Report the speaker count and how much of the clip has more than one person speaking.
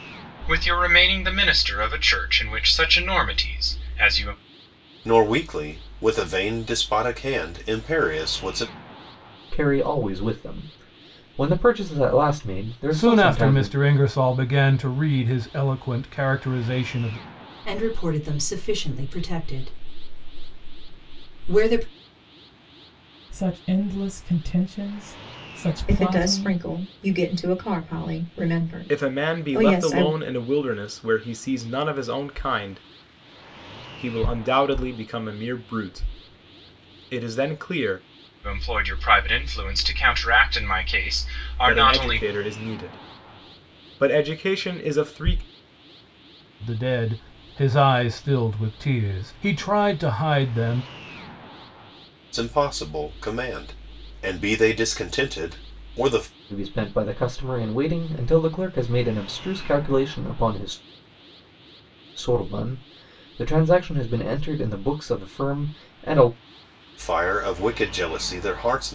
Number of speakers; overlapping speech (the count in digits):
8, about 5%